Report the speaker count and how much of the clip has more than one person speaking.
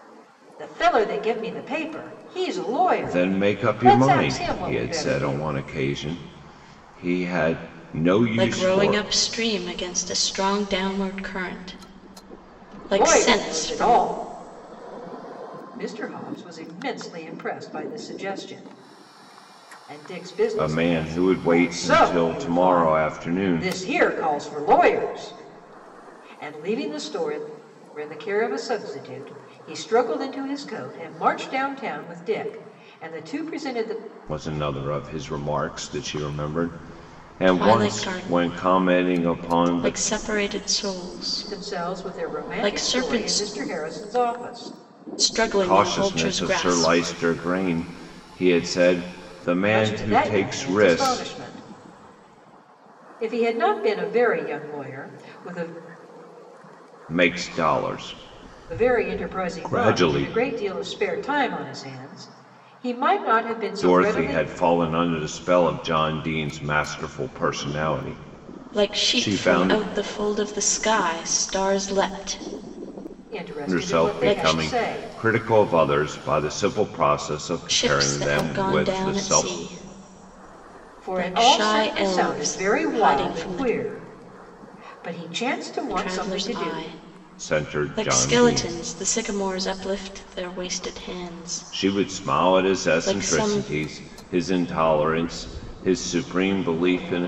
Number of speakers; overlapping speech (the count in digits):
3, about 29%